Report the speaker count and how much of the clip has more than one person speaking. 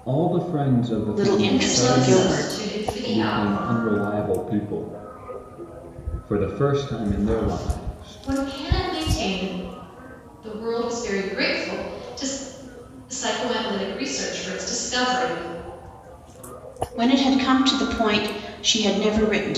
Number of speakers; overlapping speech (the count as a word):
three, about 16%